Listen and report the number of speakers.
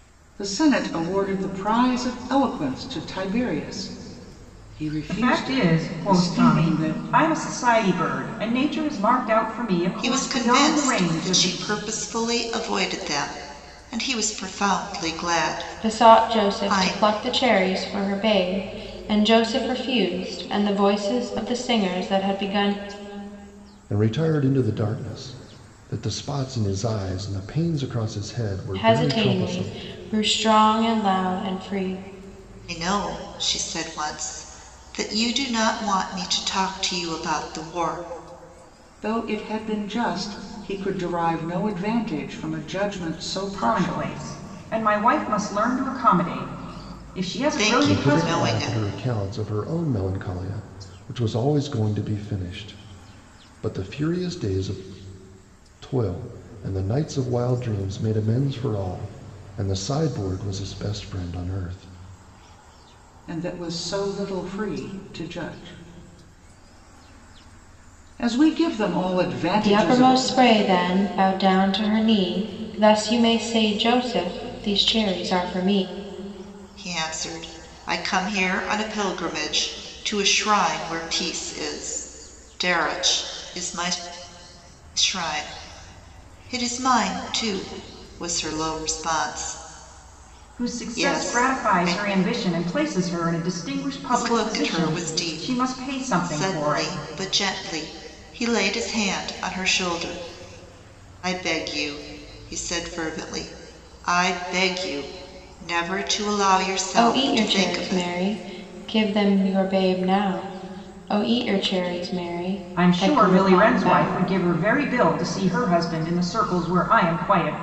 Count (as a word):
five